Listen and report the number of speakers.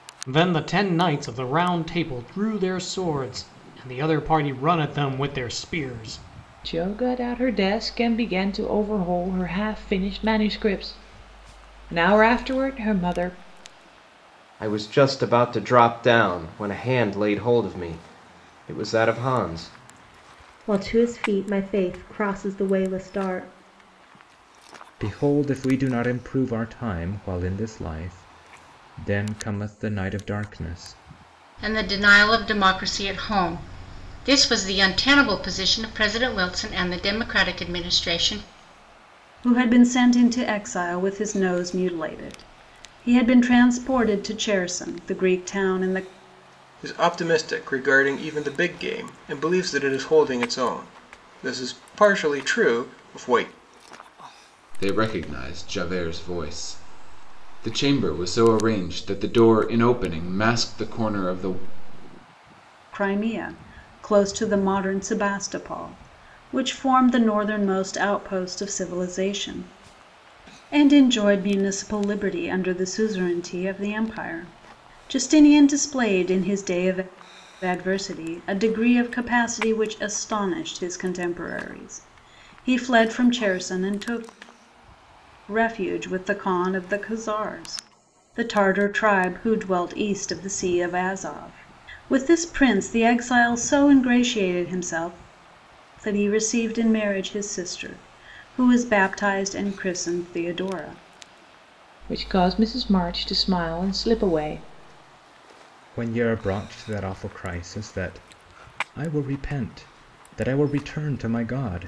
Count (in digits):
9